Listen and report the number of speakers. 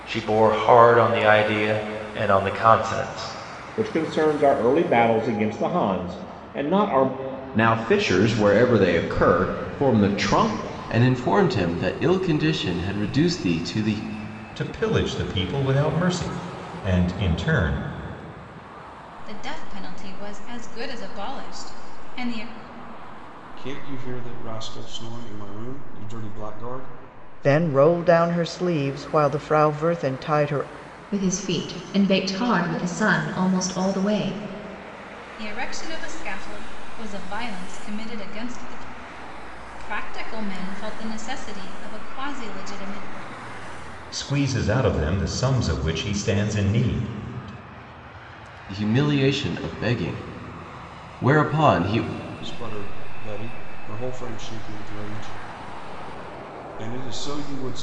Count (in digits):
9